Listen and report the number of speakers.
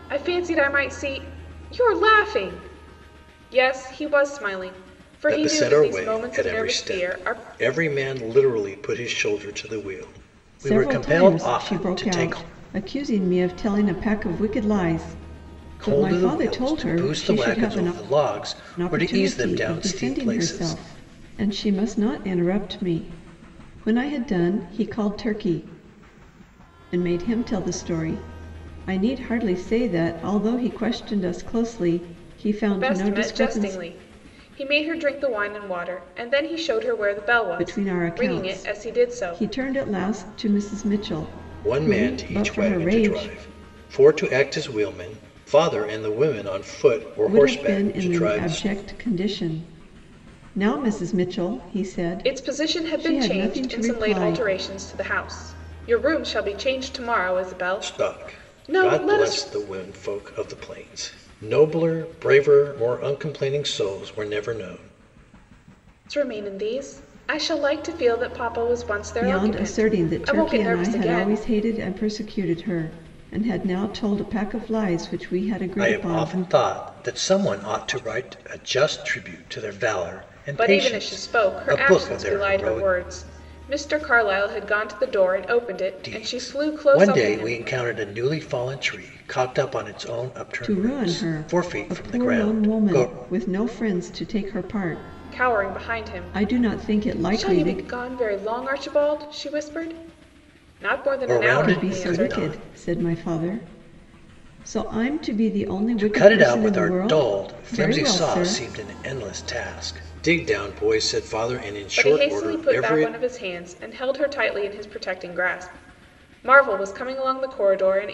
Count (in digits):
3